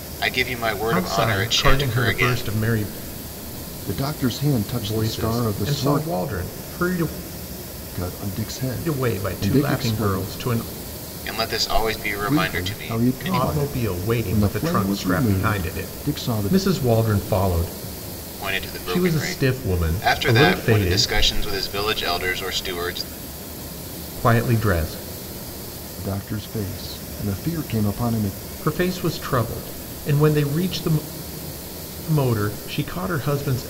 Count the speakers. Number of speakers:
3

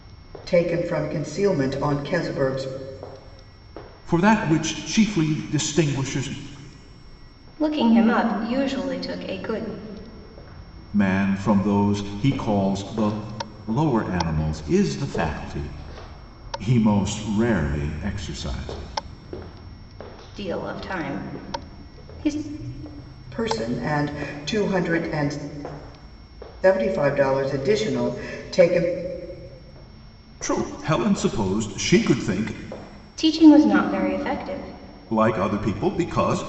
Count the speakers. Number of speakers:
3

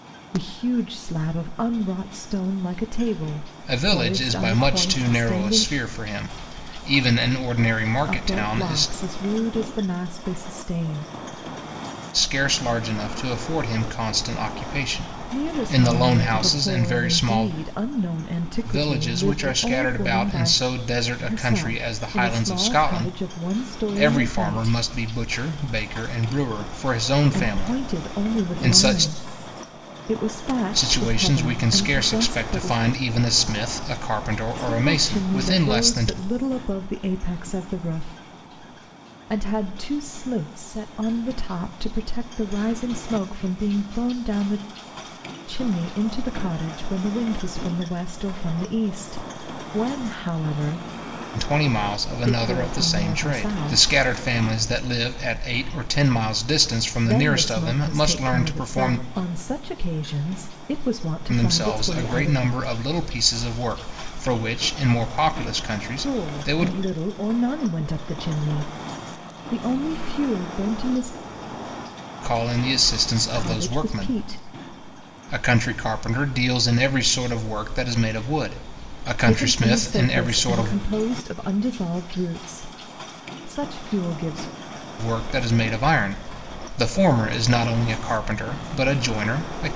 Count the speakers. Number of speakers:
2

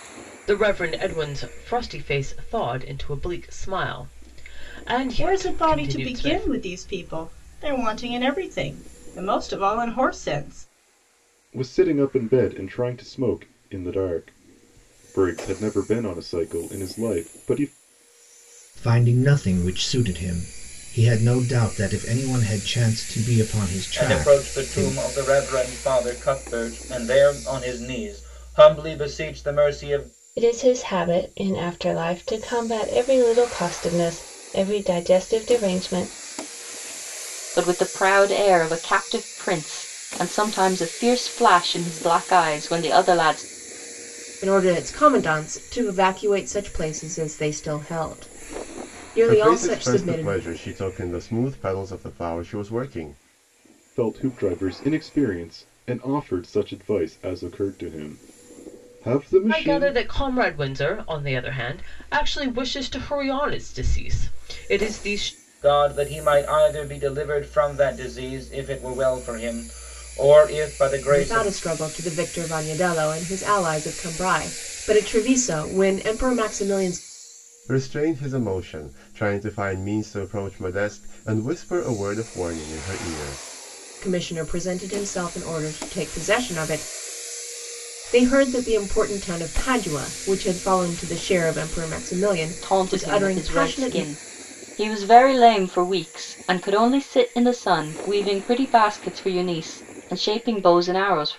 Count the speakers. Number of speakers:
9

